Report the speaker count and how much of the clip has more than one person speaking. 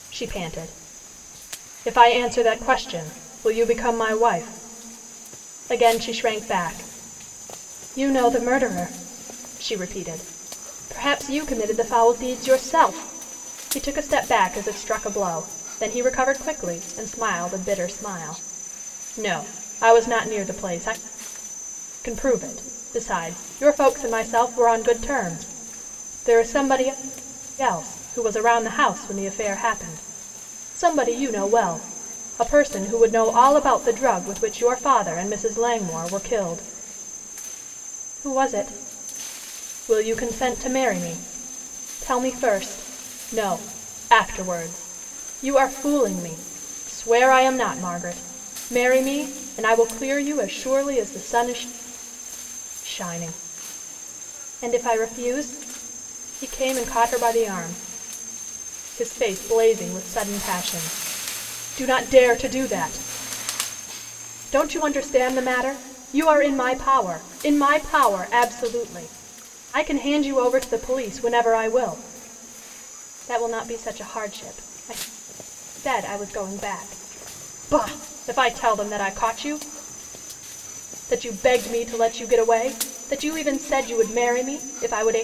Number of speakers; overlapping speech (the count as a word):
one, no overlap